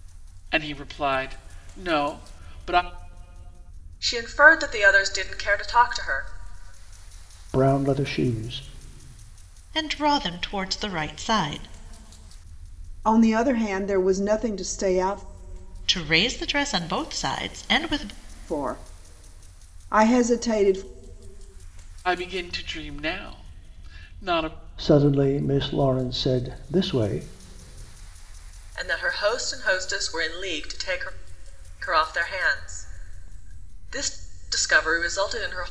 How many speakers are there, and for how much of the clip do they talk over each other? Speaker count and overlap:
five, no overlap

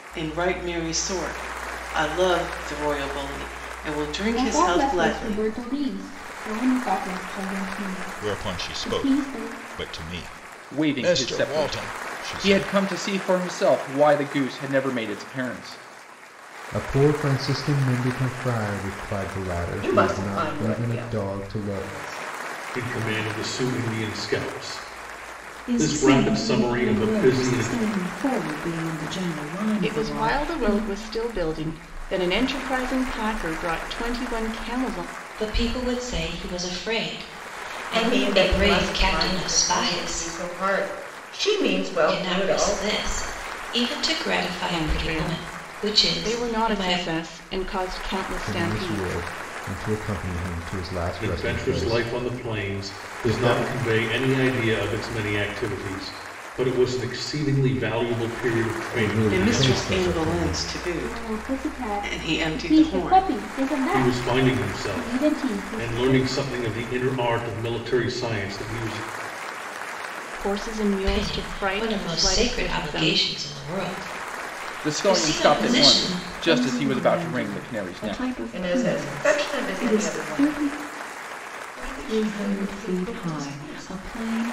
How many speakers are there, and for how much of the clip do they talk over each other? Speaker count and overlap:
ten, about 44%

